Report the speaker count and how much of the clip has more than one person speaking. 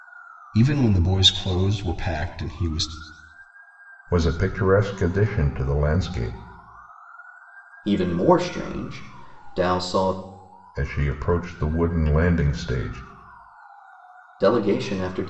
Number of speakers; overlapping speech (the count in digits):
3, no overlap